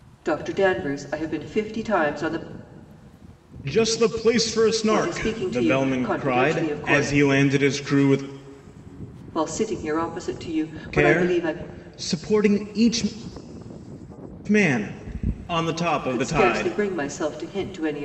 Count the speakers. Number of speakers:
two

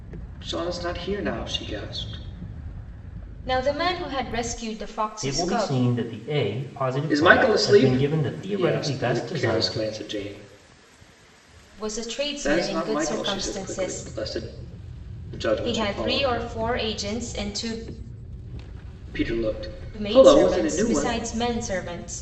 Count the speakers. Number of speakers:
three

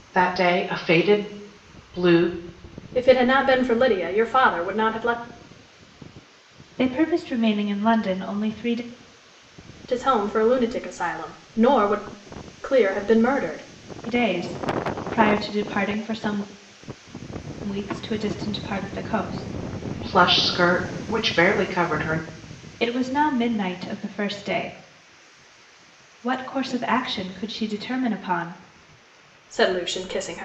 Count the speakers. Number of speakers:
three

